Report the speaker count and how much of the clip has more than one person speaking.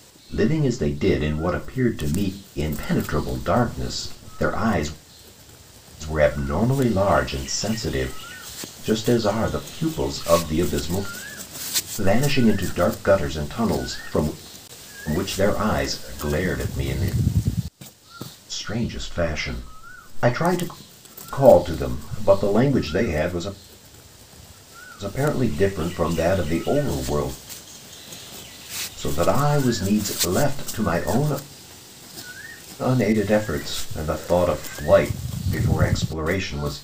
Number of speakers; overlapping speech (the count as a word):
one, no overlap